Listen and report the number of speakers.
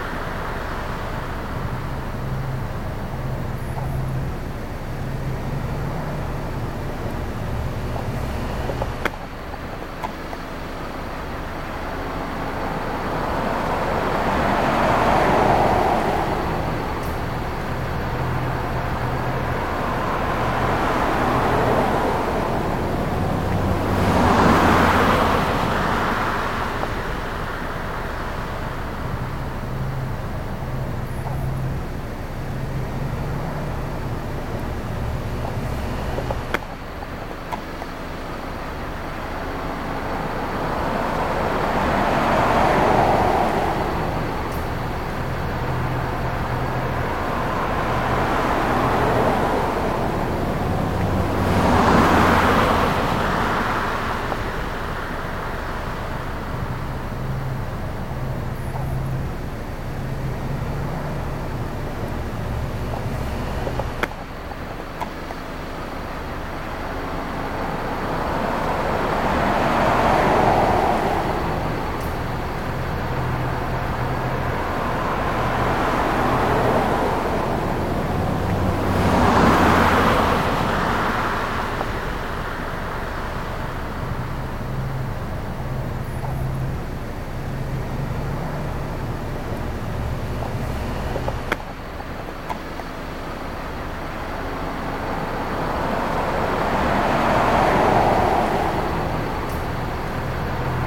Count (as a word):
zero